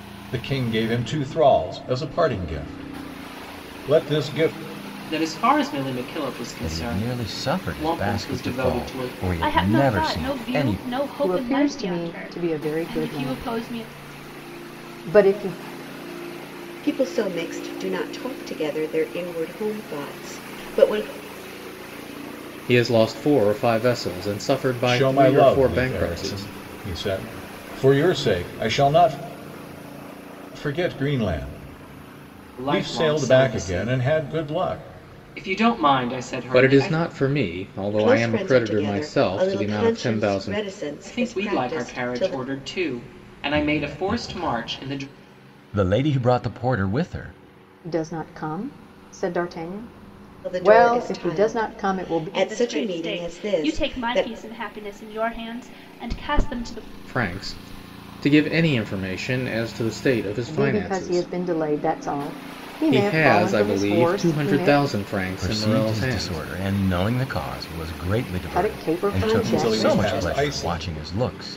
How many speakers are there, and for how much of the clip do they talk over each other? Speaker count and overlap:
seven, about 38%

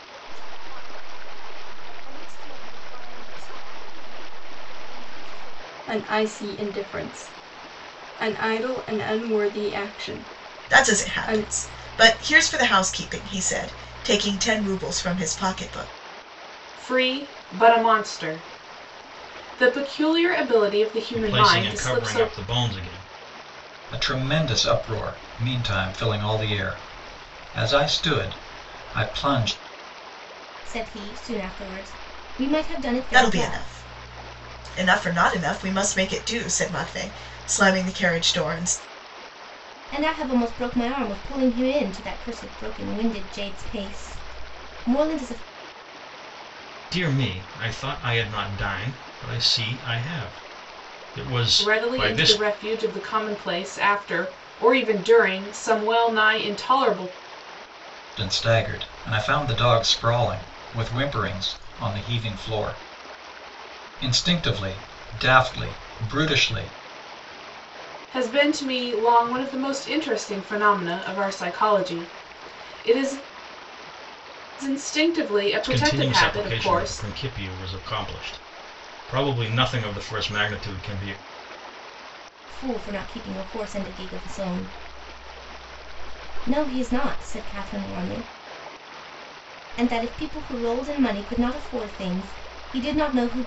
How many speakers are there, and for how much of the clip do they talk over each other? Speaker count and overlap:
seven, about 5%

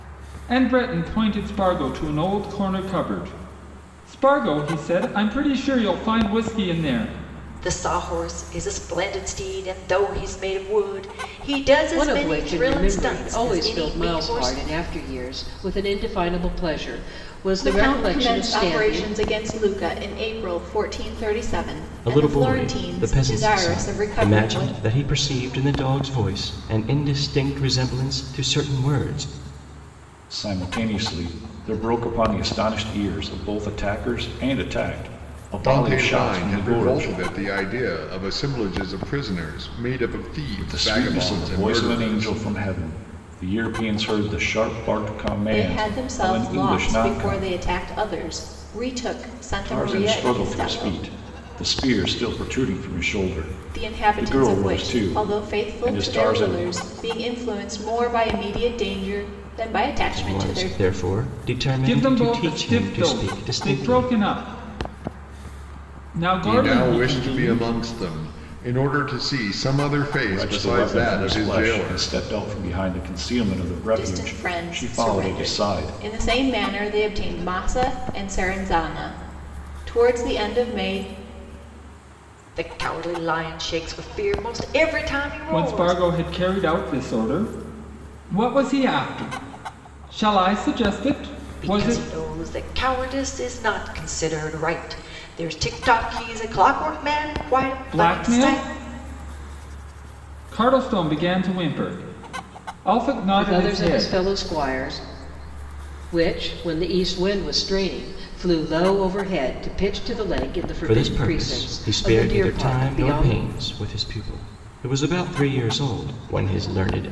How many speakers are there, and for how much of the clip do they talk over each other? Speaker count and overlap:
seven, about 26%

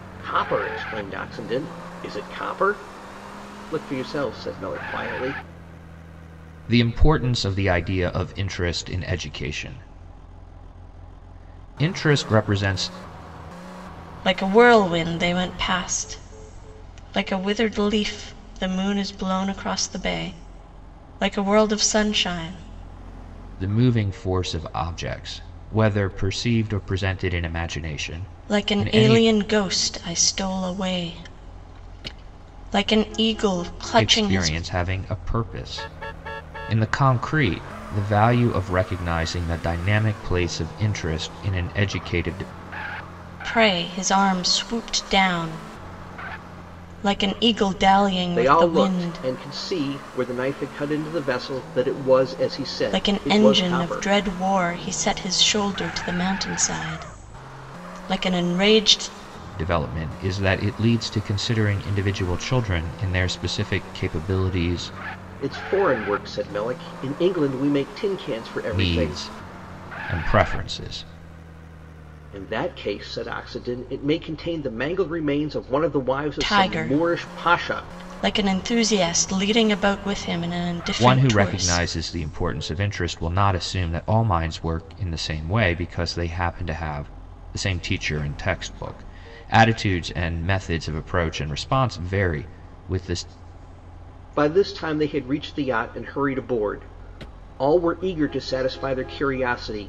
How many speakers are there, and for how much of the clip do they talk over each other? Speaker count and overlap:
three, about 7%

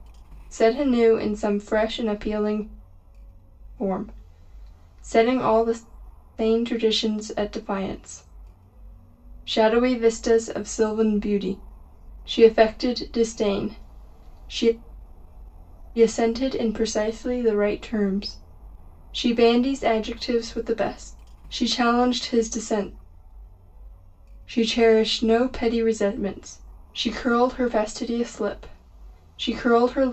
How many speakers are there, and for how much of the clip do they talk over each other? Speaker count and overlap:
one, no overlap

